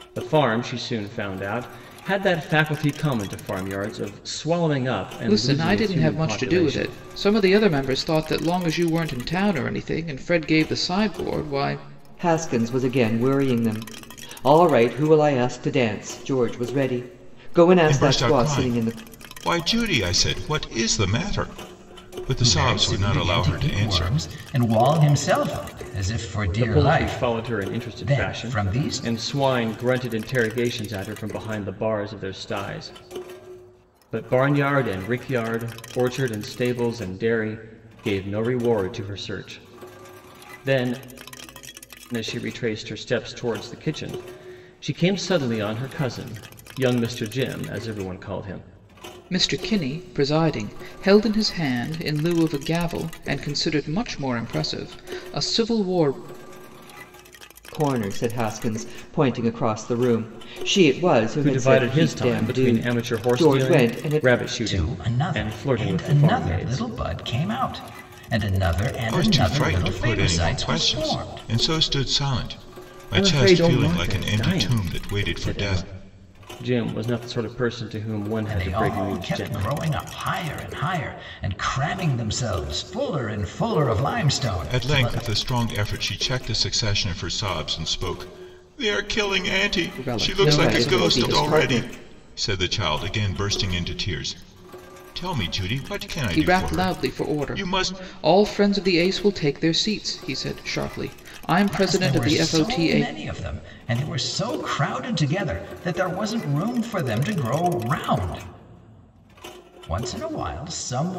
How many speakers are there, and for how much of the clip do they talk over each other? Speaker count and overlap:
5, about 22%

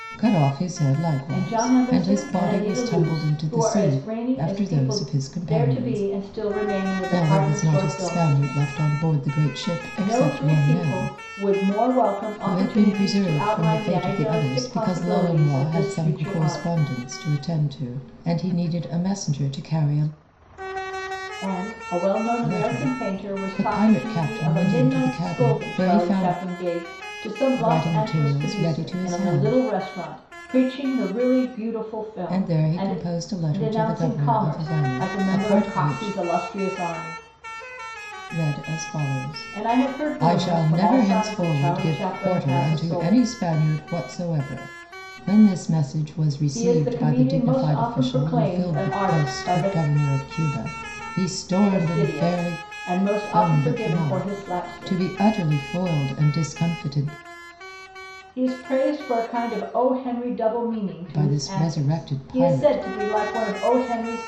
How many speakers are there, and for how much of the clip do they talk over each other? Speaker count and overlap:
2, about 52%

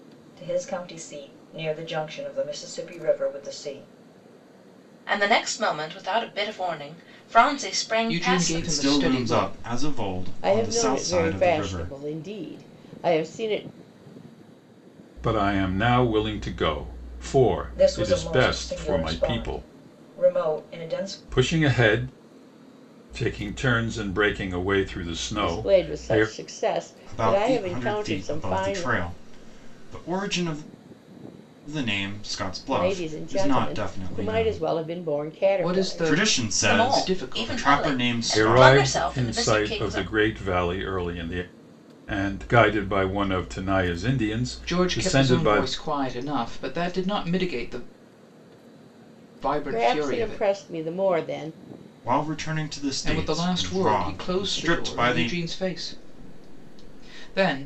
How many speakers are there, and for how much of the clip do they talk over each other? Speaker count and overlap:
6, about 35%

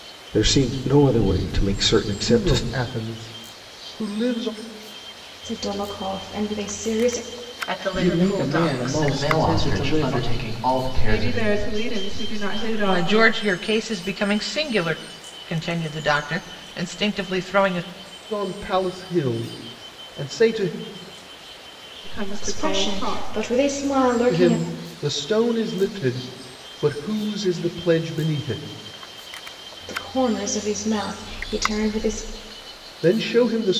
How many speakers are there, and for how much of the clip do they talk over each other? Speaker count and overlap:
8, about 15%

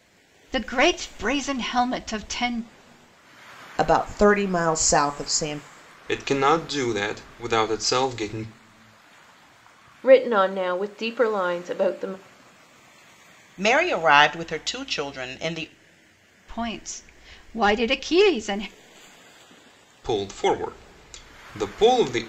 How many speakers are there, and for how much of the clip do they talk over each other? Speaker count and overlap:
5, no overlap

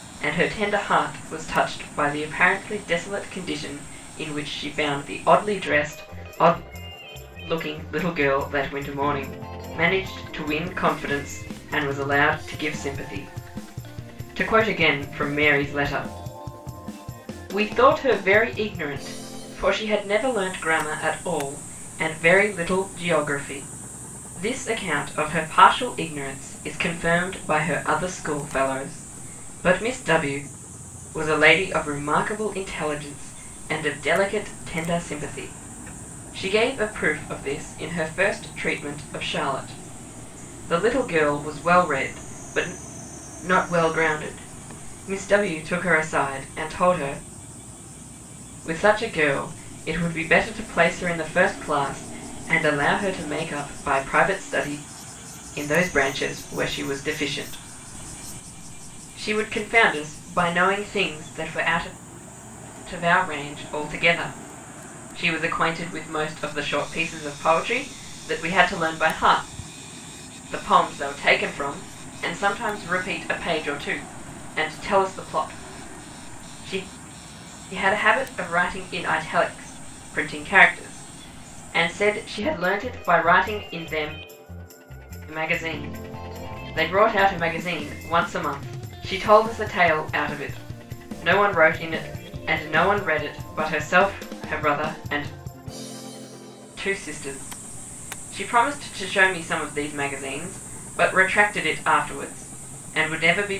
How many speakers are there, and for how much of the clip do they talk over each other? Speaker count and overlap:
1, no overlap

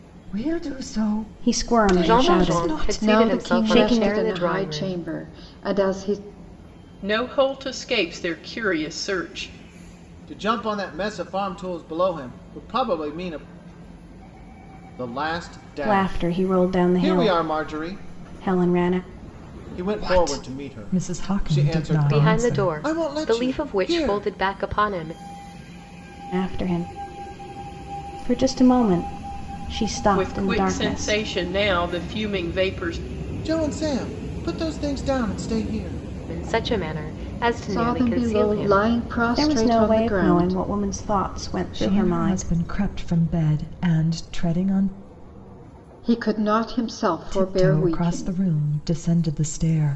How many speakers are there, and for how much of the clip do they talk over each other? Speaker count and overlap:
6, about 30%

